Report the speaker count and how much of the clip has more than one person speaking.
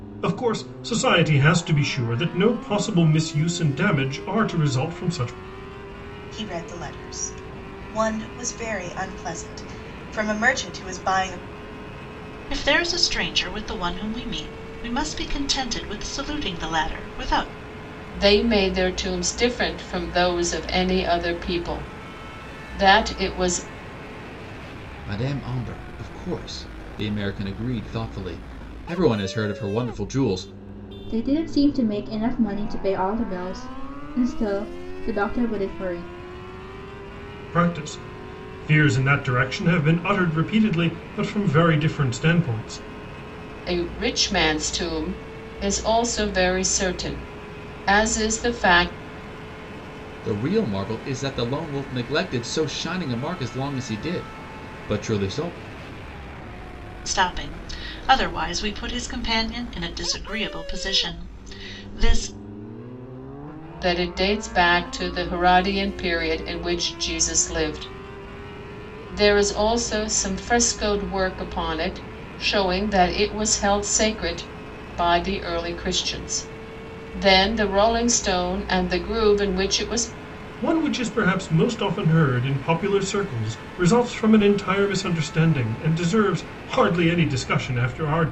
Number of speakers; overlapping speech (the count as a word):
six, no overlap